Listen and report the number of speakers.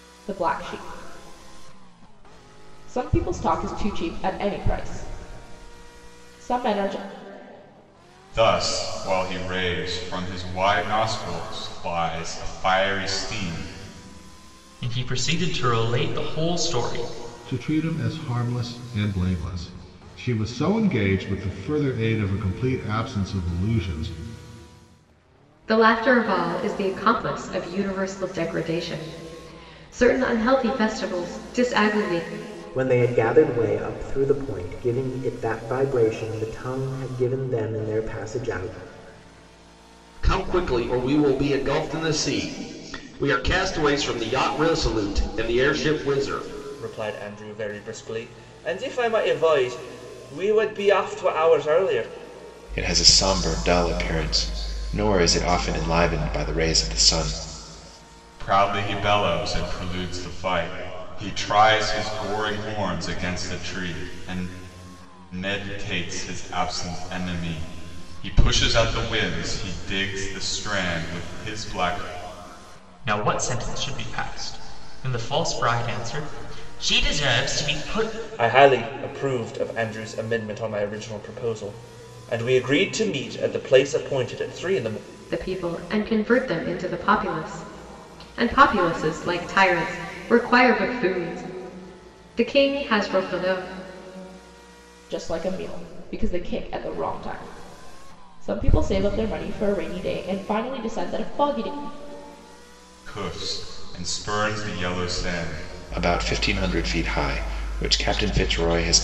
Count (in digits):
9